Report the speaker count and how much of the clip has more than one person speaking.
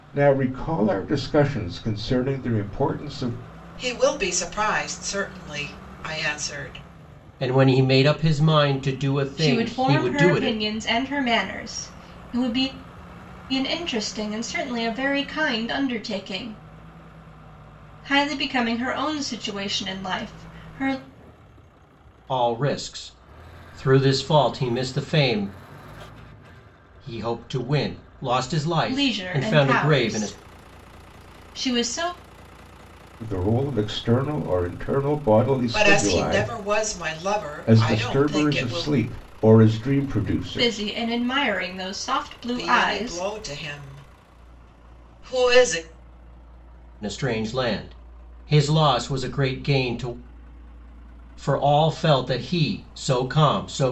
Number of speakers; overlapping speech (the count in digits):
4, about 11%